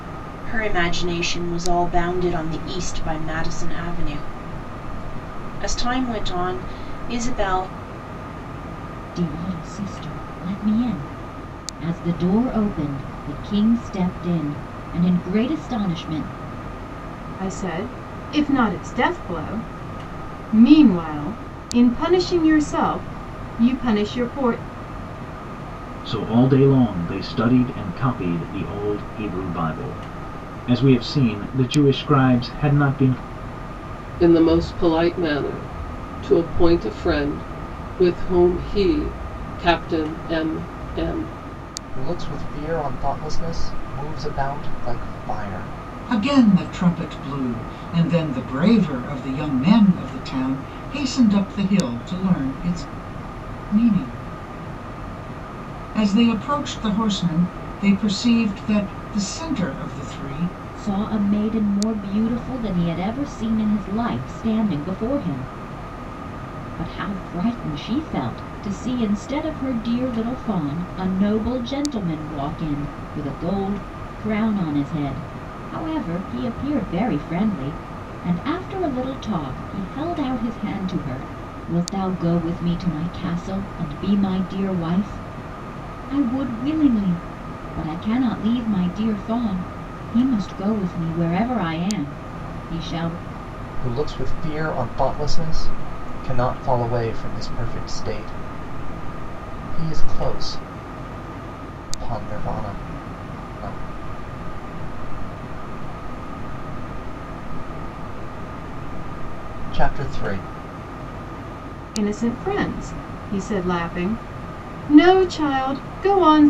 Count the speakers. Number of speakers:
seven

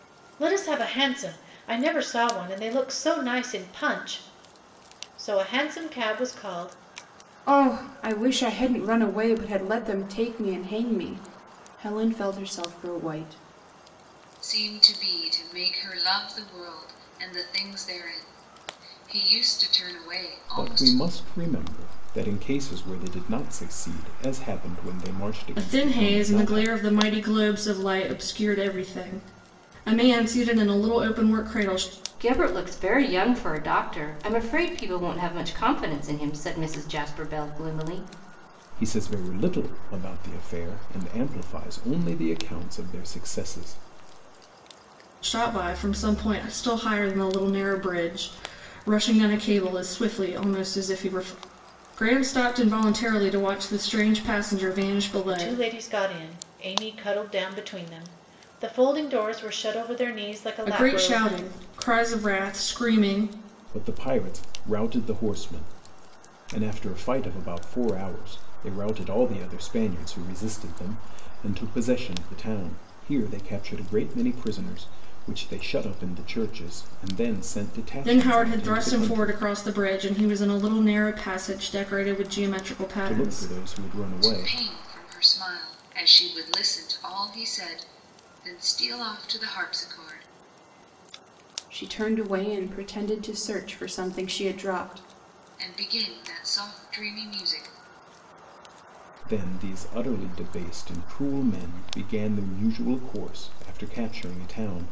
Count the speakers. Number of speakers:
six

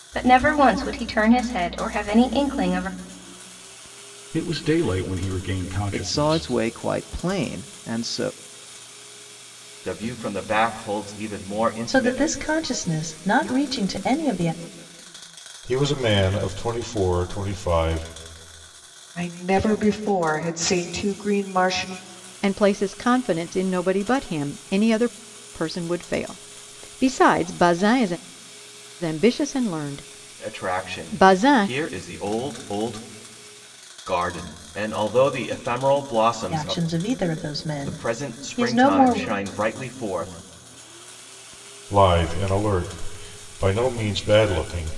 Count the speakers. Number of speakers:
eight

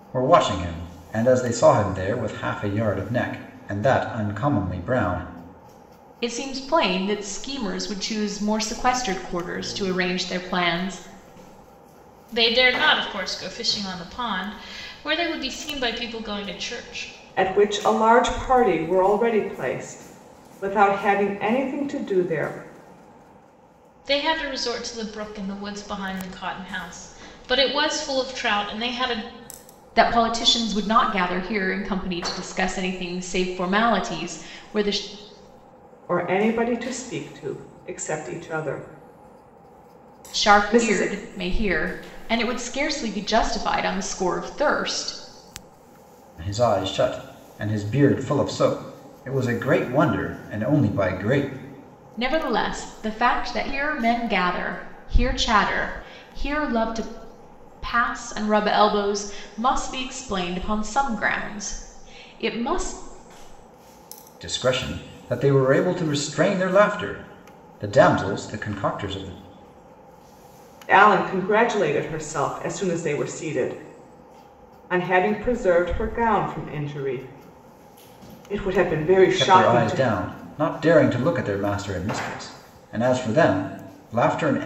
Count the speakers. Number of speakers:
four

